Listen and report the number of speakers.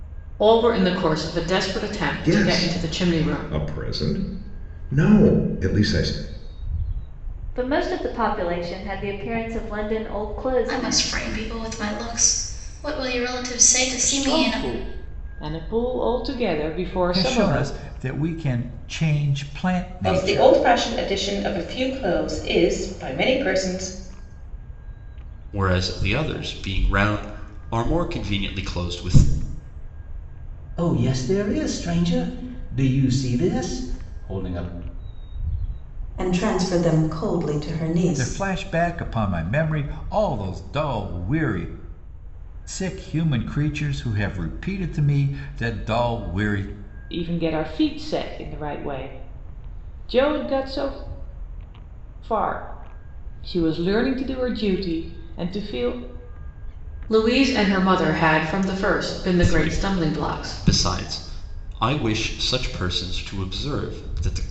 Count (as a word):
ten